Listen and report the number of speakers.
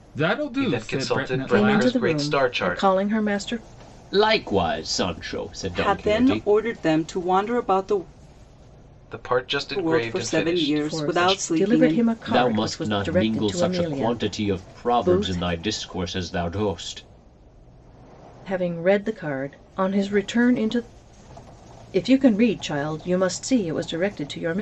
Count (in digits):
5